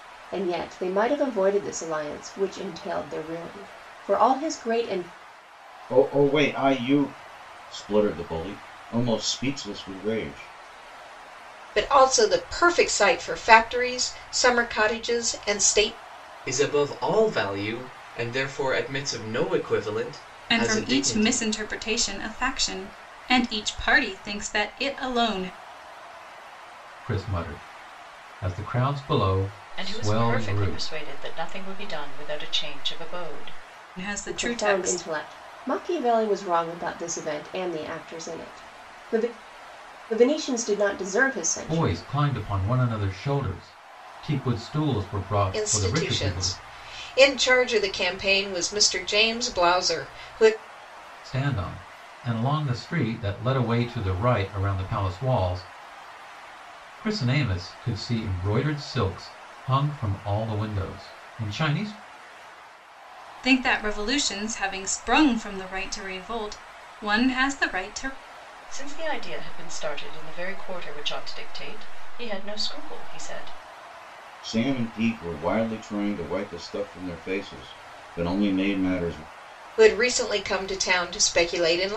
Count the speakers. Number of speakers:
7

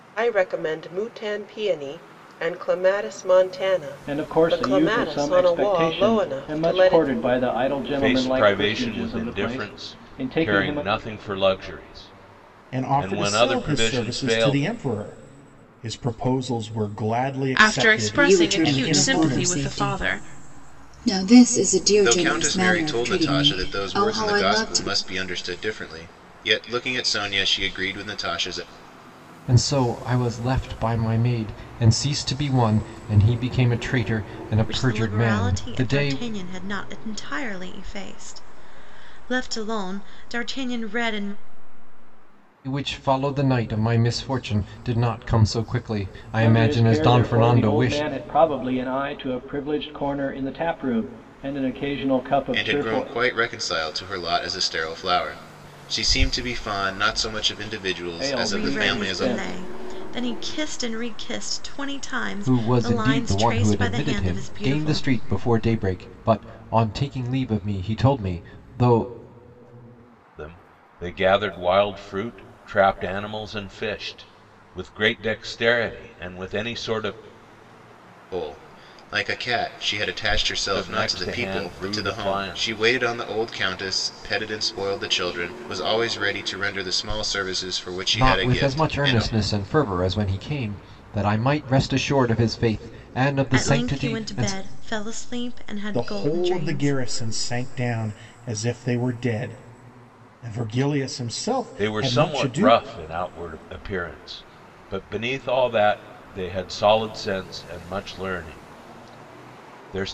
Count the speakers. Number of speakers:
9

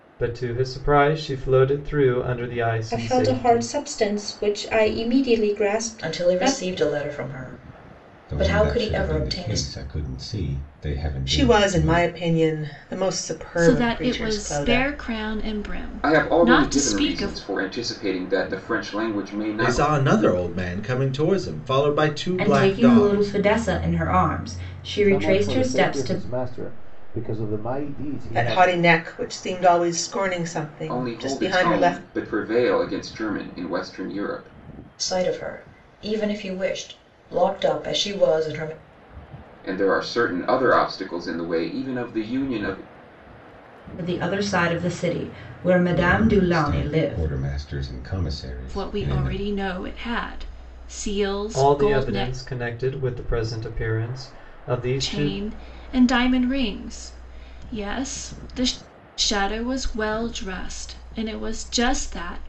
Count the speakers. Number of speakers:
10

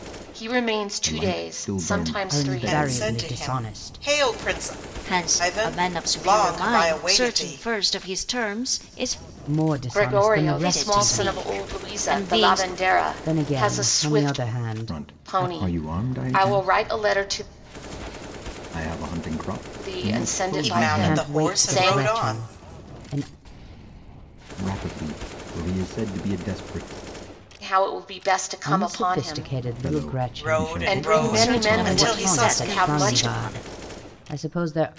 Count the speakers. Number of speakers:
5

